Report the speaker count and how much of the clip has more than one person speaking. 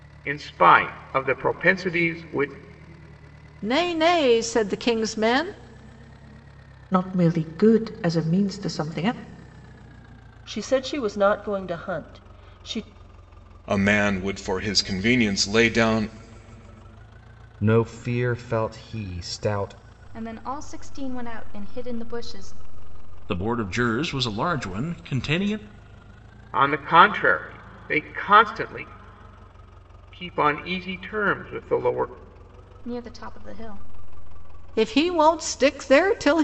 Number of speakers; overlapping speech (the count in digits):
8, no overlap